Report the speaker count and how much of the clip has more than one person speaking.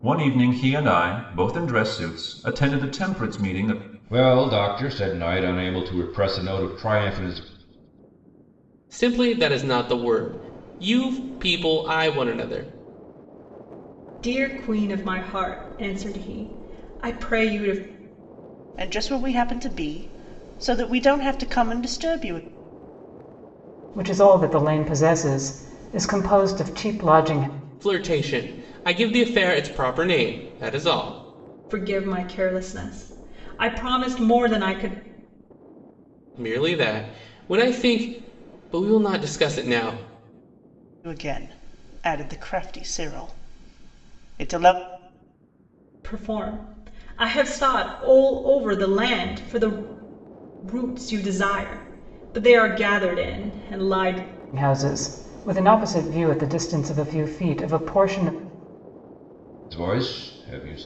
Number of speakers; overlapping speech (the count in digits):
6, no overlap